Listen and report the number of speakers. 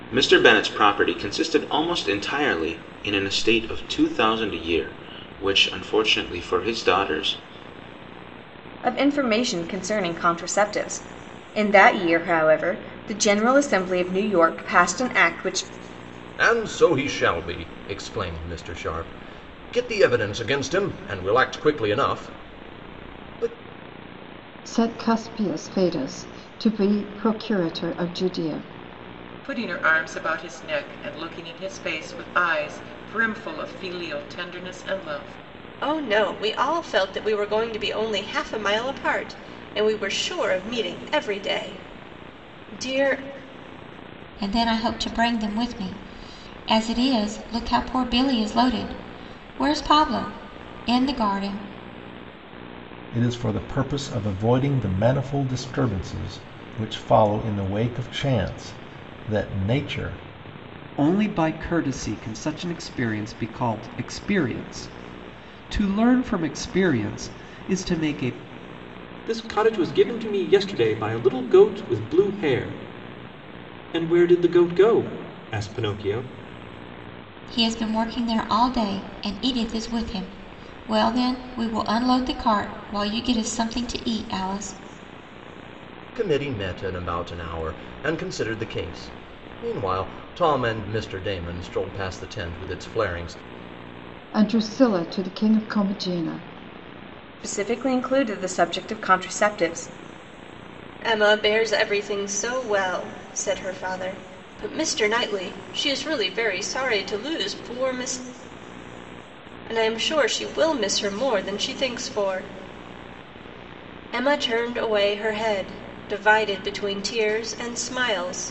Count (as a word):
ten